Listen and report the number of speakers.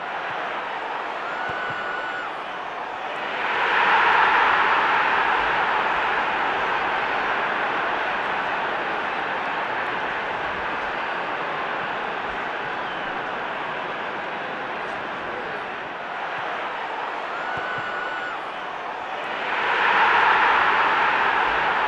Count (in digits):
0